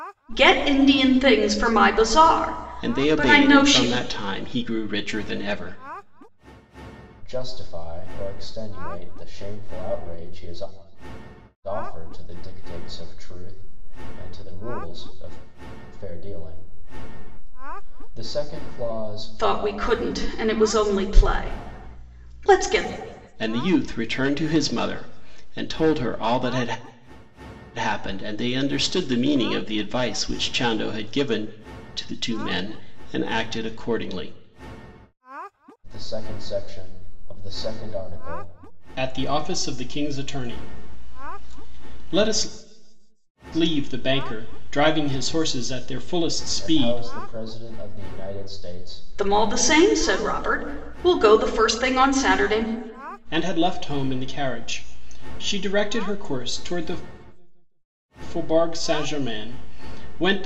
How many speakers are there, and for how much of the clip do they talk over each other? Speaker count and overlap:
three, about 4%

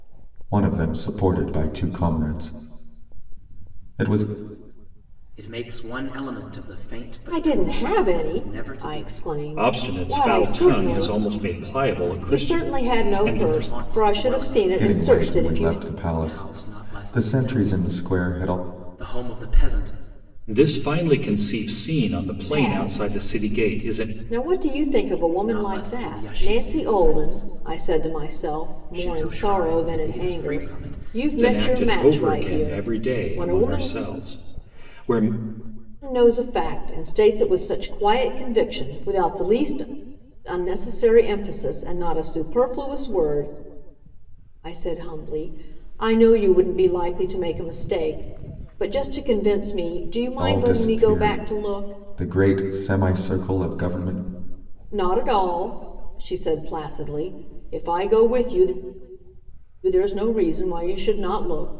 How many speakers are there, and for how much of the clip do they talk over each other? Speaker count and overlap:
four, about 33%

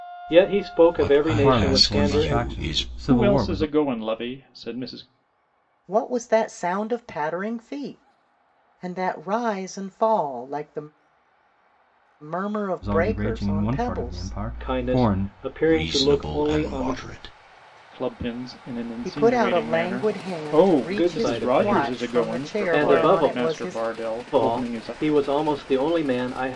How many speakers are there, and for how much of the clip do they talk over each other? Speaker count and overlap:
five, about 43%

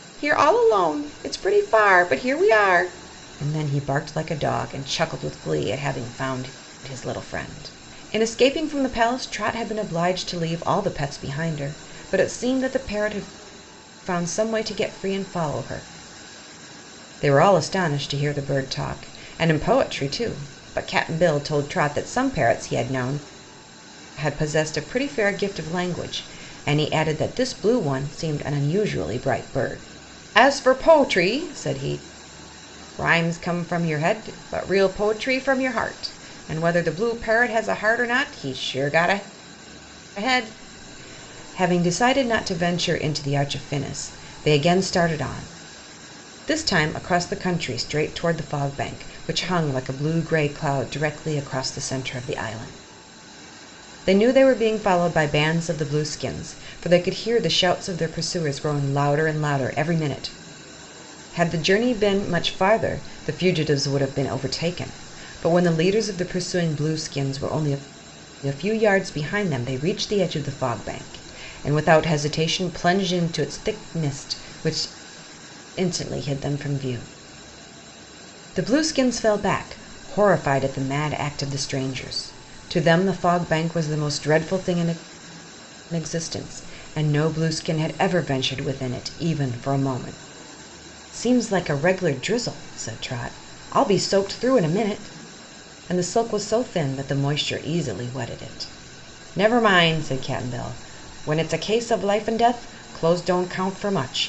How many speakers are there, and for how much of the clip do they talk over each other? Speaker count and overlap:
one, no overlap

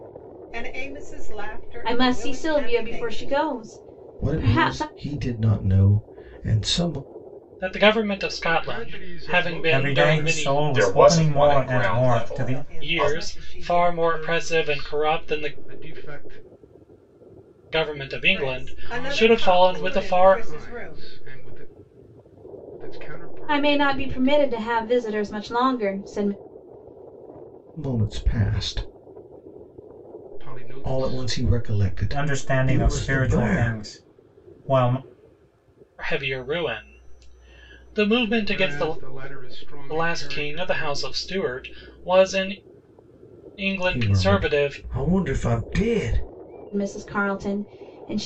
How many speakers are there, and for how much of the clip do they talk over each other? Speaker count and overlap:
seven, about 39%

